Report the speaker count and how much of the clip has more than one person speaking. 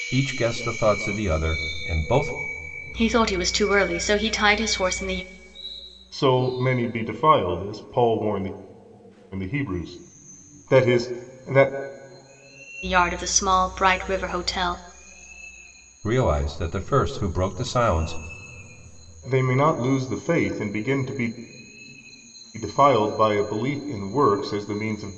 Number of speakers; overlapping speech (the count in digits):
3, no overlap